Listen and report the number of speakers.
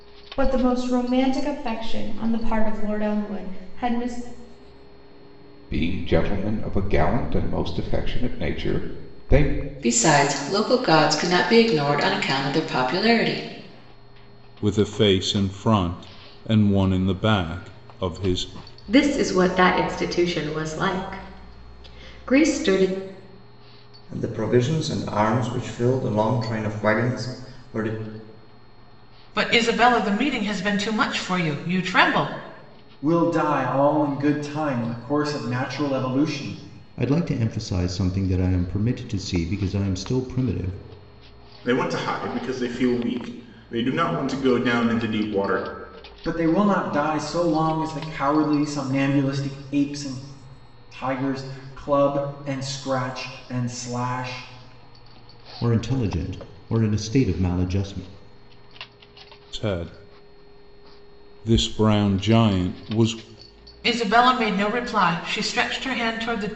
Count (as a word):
ten